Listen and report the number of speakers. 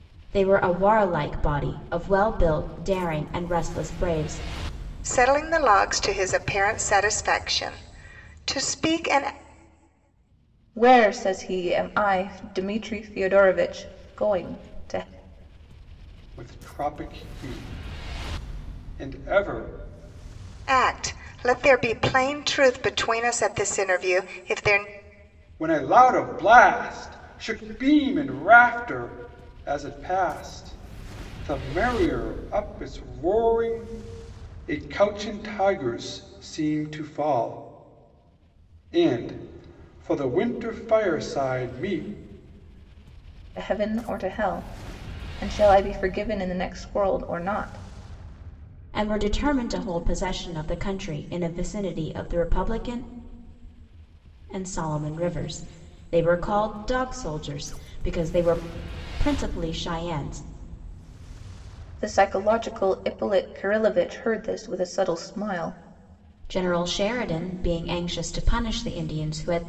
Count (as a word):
four